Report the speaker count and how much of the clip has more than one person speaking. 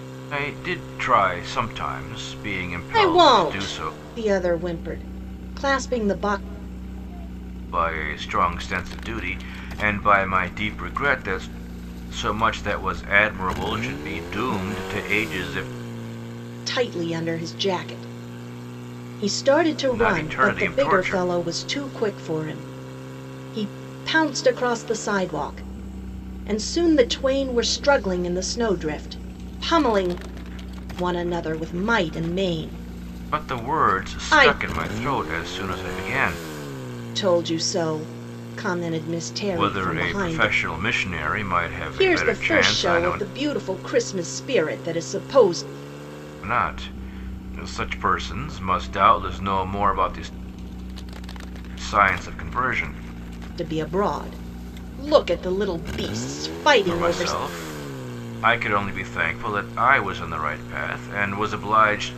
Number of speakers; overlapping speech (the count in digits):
2, about 11%